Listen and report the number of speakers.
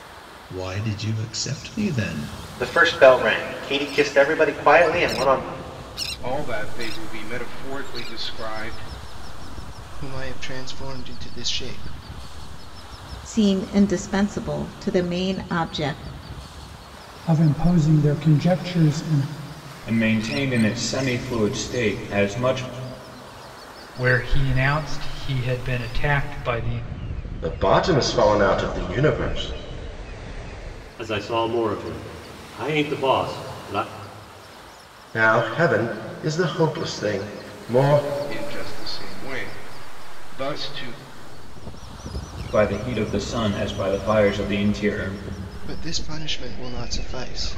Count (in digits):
10